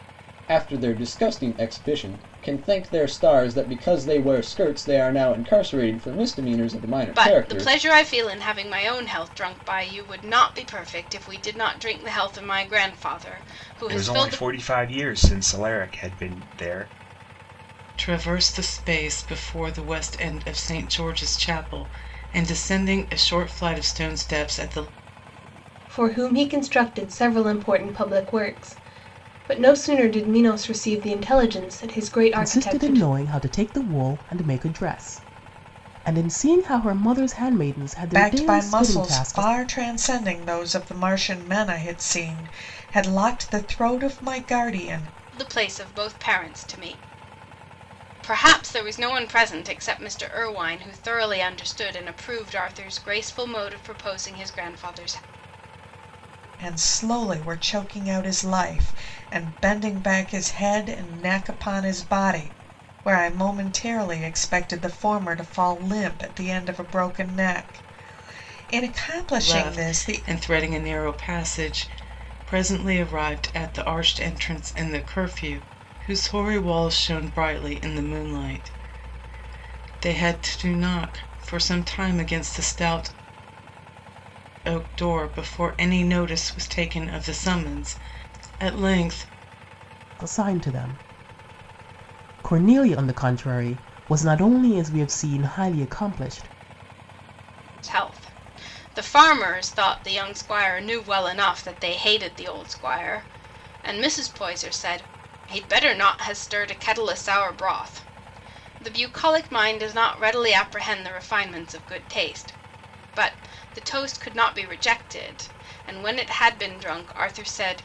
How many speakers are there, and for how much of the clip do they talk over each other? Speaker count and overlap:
seven, about 4%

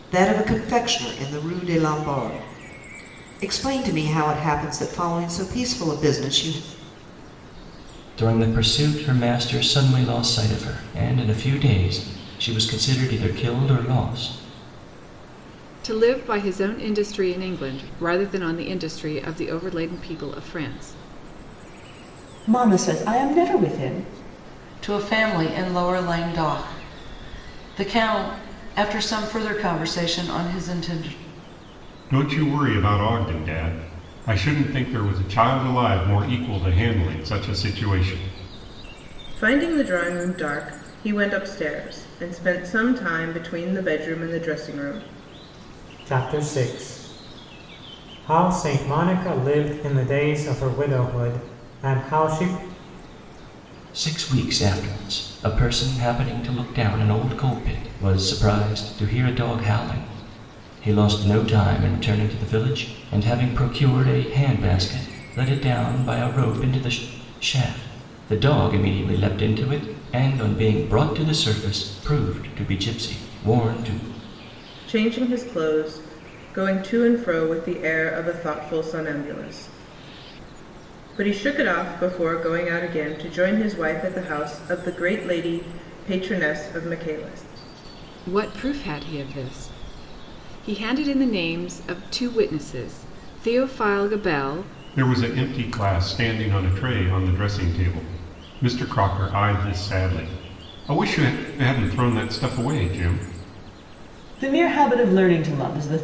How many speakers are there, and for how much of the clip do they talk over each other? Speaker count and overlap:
eight, no overlap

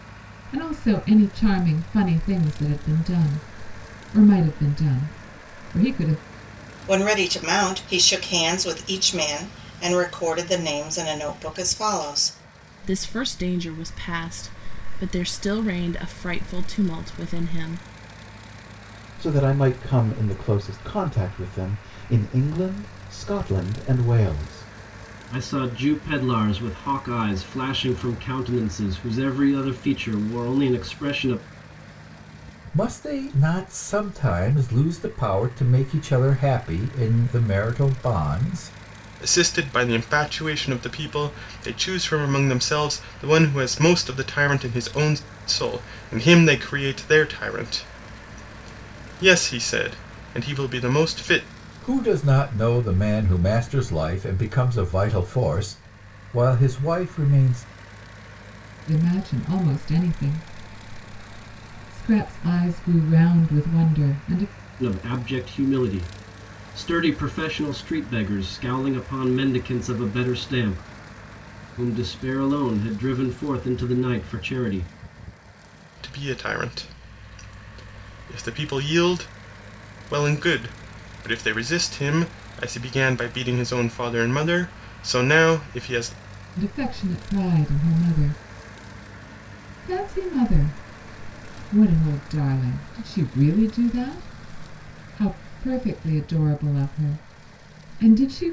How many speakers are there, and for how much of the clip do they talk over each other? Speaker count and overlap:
seven, no overlap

